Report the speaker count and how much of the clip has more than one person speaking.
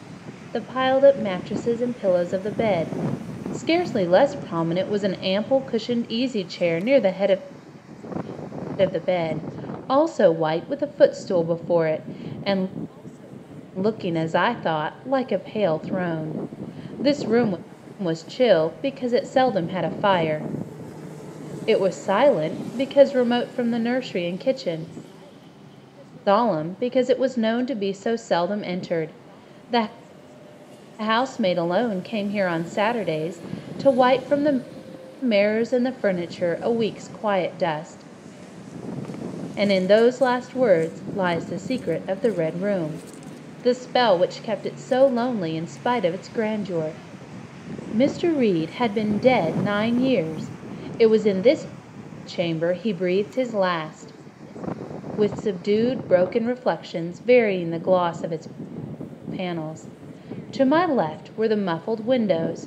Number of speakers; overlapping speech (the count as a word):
one, no overlap